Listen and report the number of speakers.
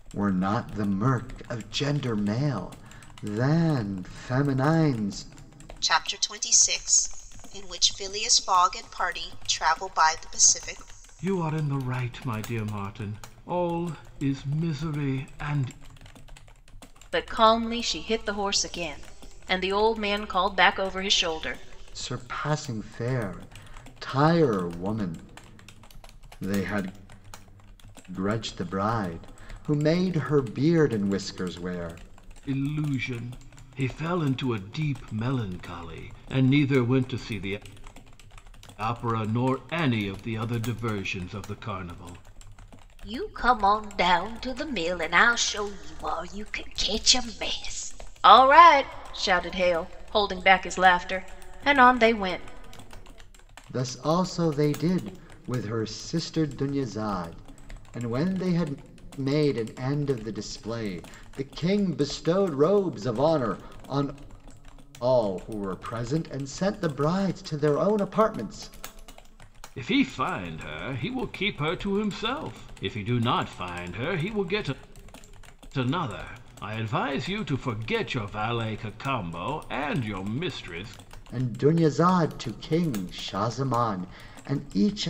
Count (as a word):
four